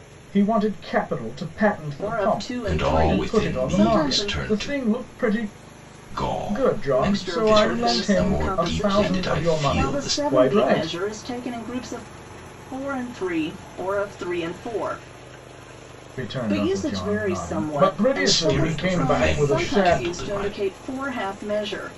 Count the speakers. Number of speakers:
three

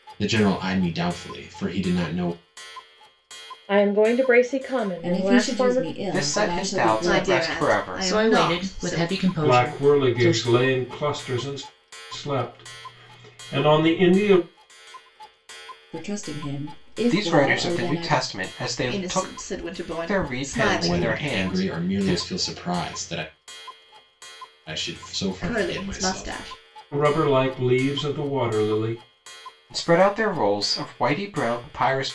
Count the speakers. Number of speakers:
seven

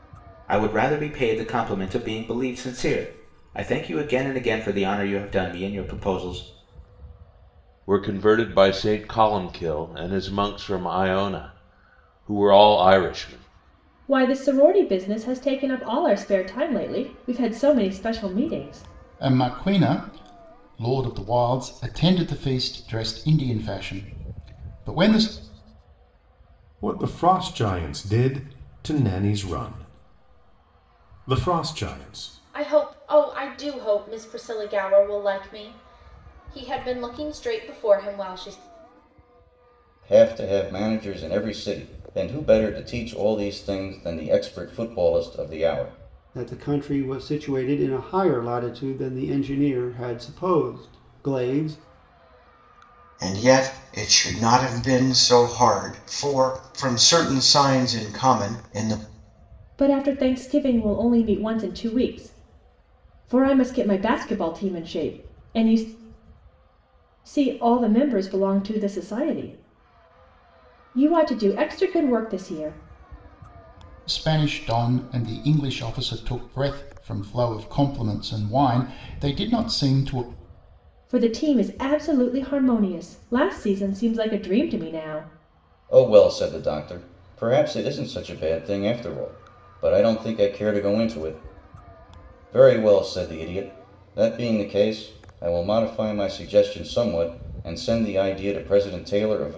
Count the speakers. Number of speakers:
nine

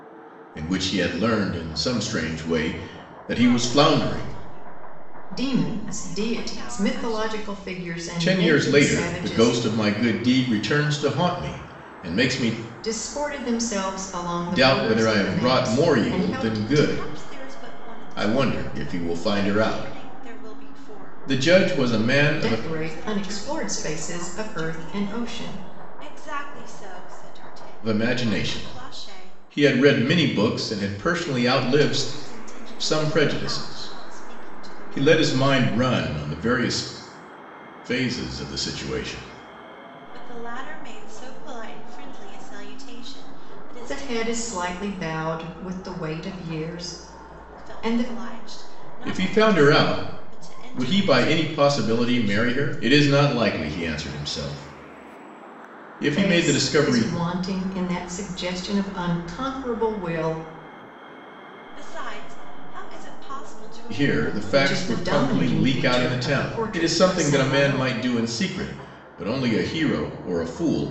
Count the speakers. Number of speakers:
three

